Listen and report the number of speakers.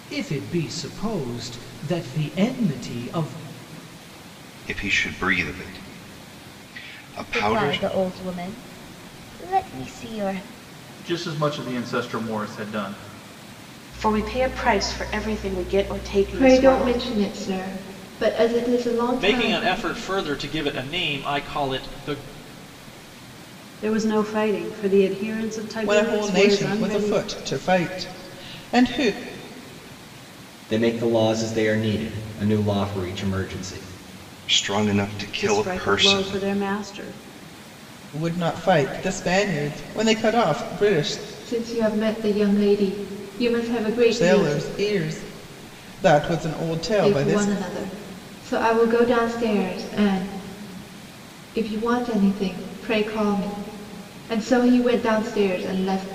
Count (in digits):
10